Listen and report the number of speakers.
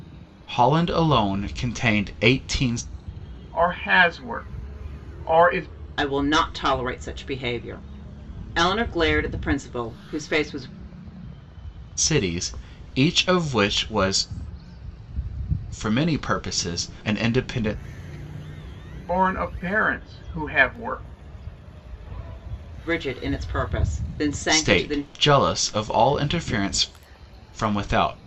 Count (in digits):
3